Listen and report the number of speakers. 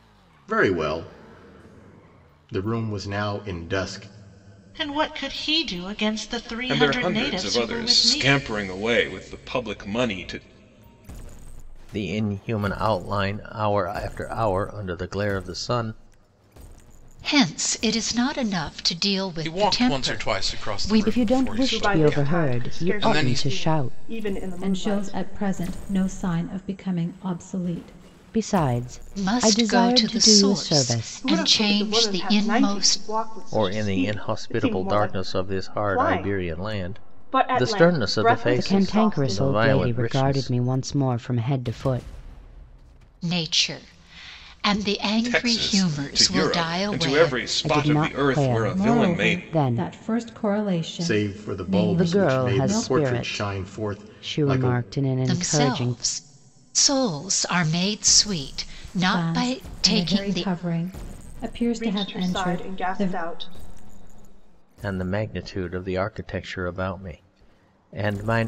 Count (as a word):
nine